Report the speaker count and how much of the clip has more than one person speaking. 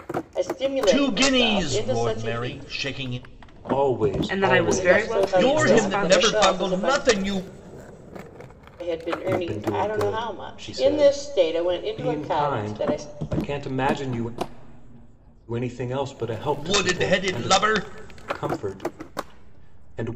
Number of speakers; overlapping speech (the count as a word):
four, about 44%